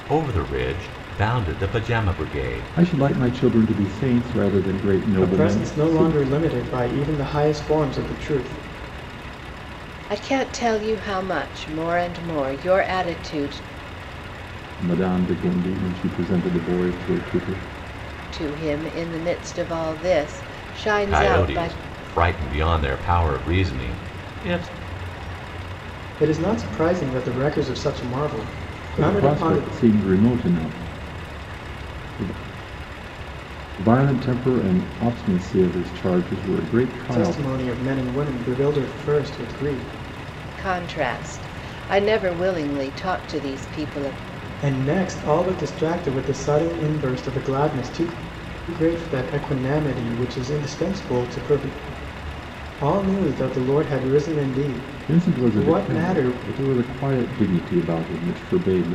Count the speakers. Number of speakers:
4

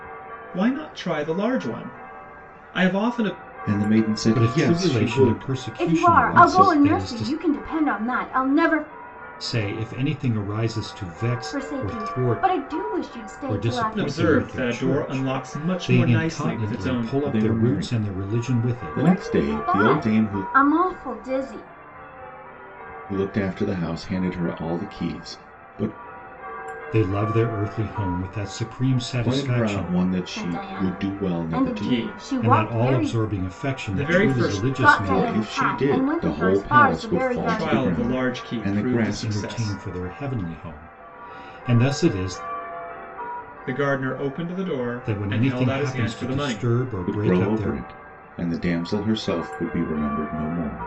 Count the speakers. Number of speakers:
4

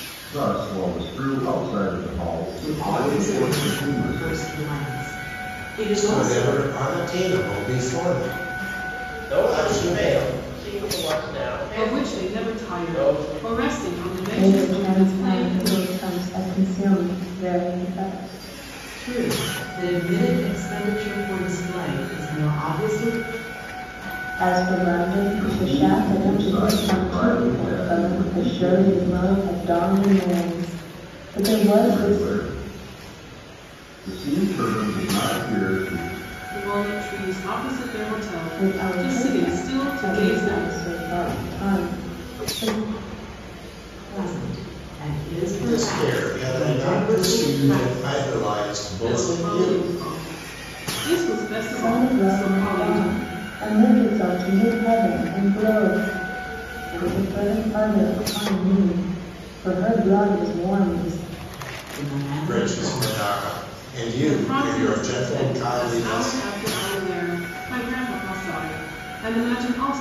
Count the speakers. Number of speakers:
6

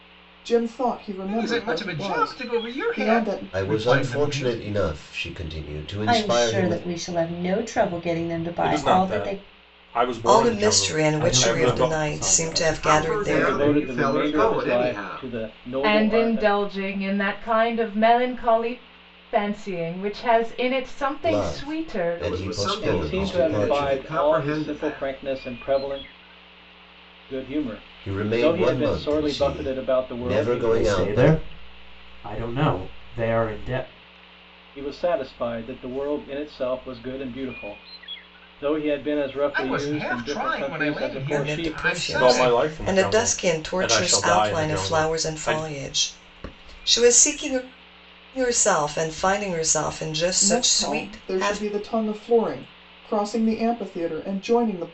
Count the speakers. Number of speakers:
10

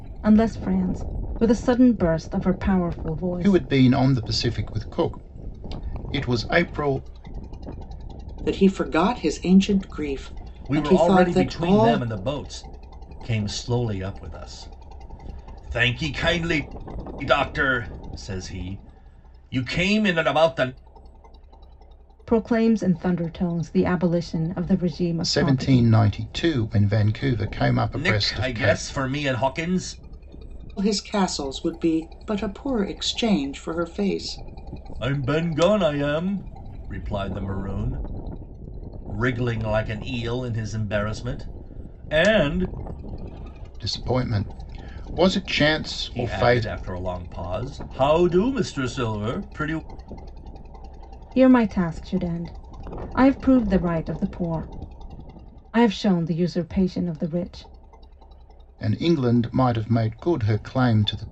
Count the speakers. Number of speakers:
4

